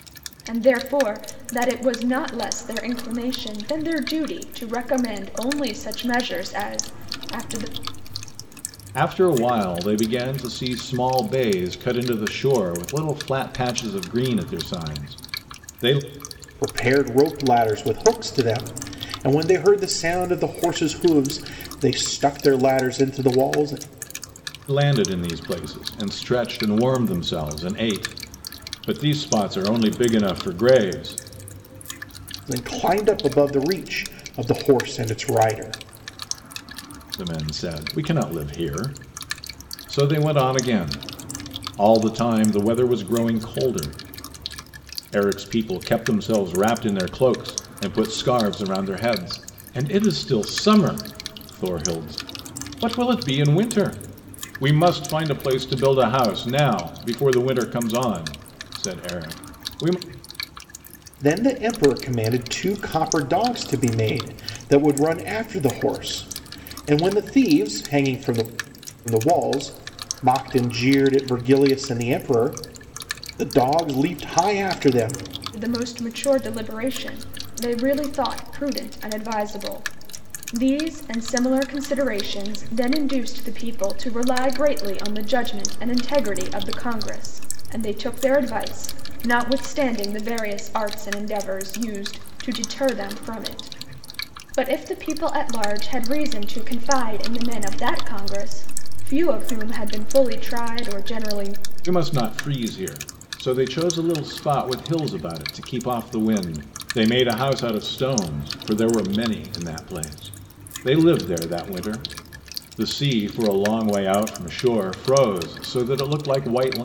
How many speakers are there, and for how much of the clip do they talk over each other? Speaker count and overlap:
3, no overlap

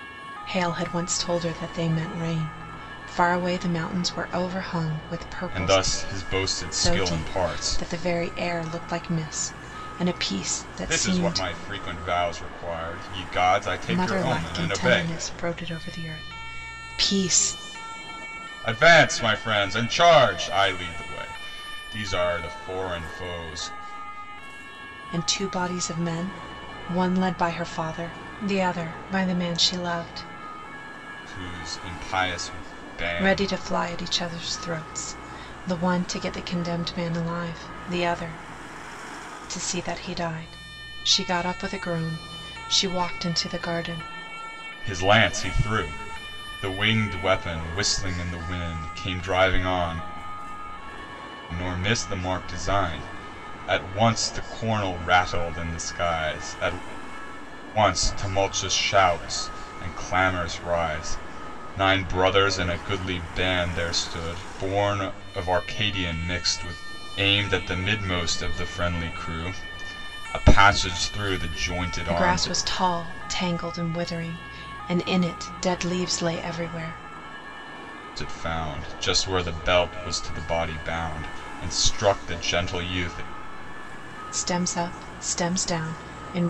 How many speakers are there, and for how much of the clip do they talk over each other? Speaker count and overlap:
2, about 5%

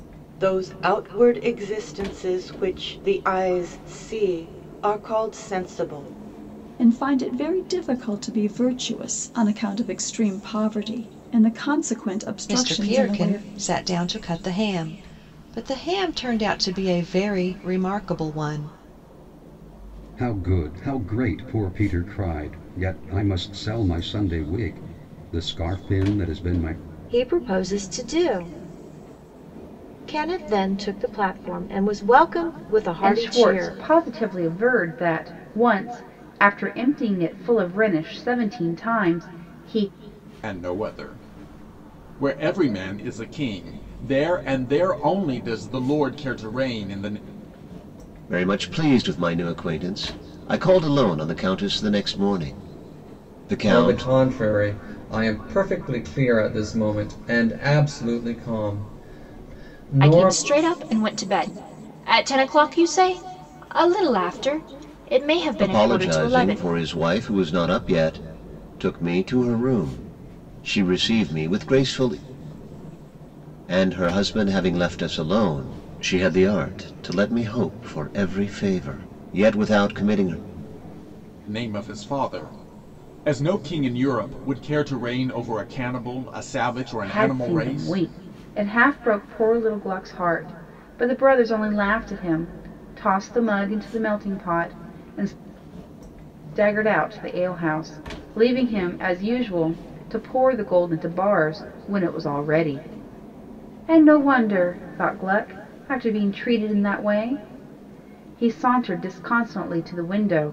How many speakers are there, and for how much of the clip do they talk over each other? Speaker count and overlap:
10, about 4%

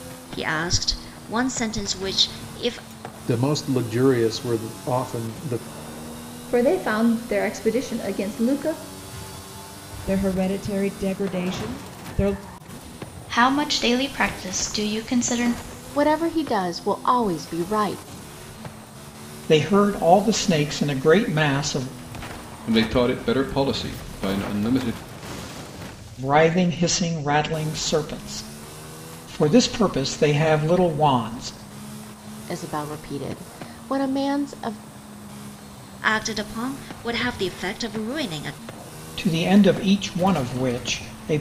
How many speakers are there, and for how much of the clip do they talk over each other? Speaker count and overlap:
8, no overlap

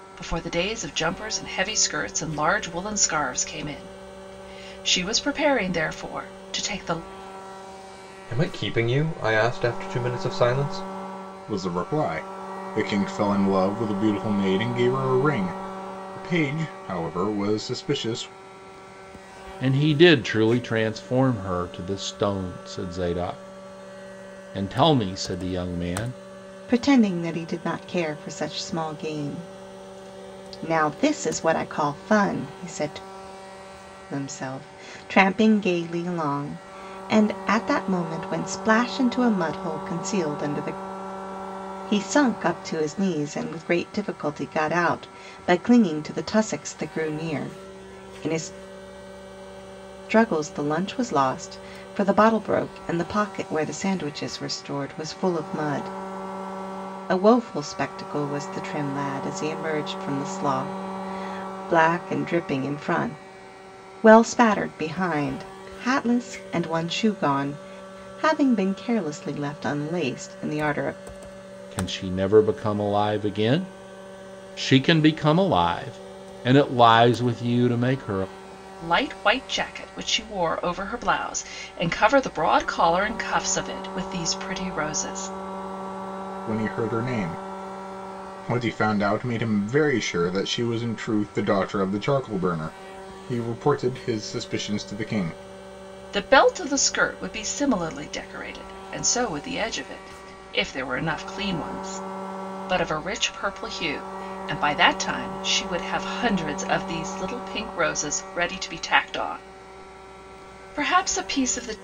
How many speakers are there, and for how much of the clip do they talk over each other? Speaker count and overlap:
5, no overlap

